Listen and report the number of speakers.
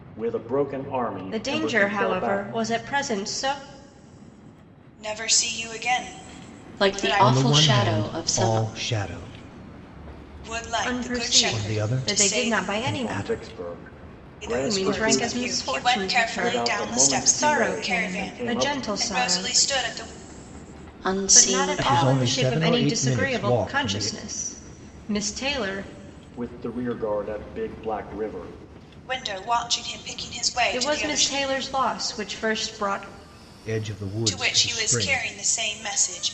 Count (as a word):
five